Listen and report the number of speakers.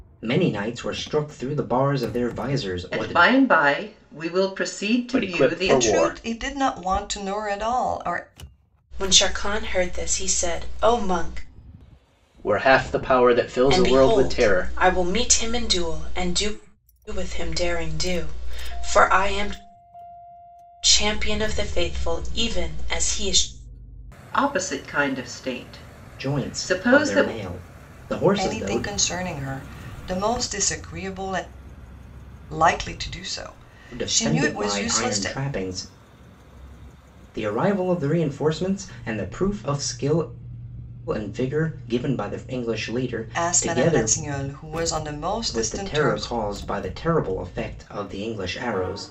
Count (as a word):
five